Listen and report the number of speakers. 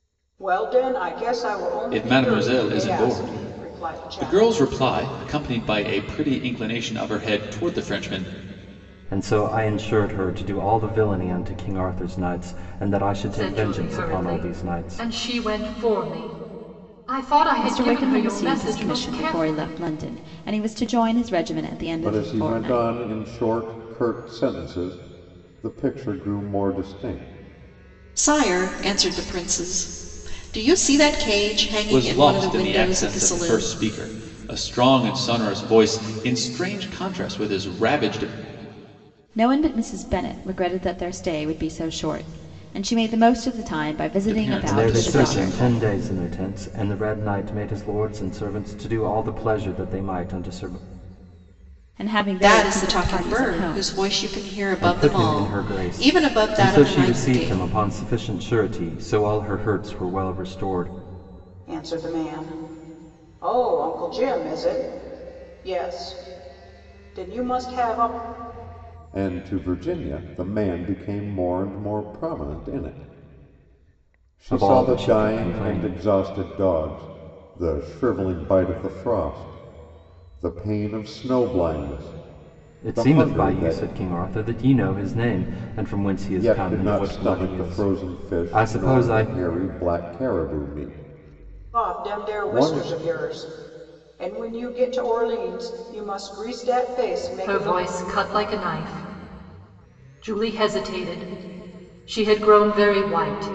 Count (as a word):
seven